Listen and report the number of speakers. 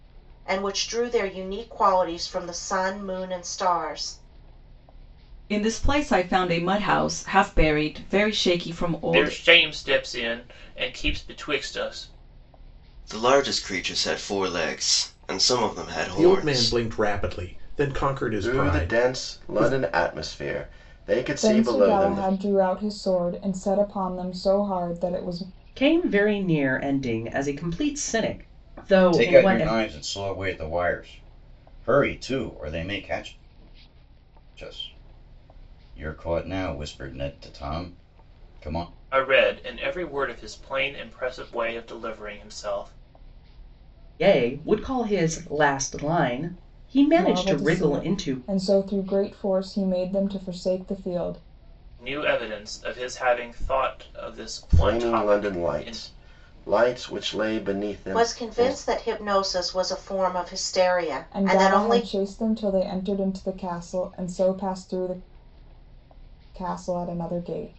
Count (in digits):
9